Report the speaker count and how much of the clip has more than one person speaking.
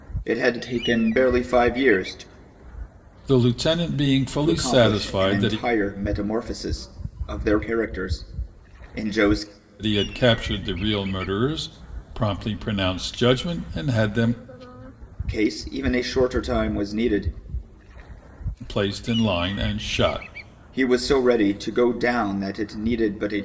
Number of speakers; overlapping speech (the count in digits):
2, about 5%